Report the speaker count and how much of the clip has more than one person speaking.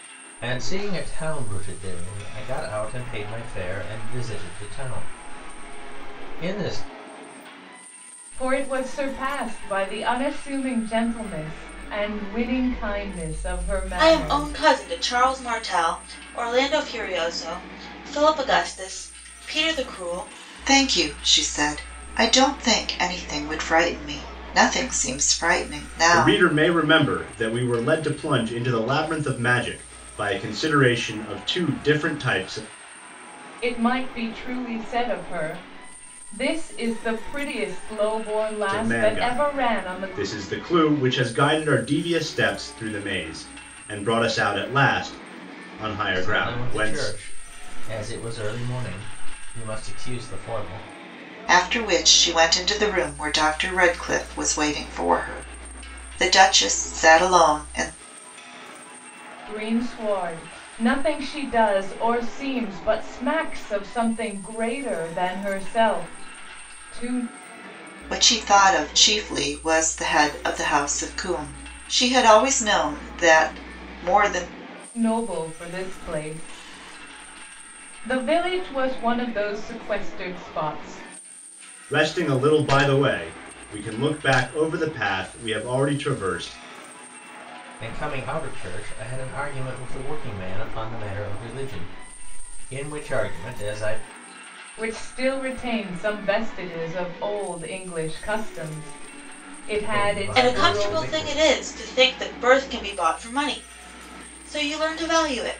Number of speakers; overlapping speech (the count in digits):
5, about 5%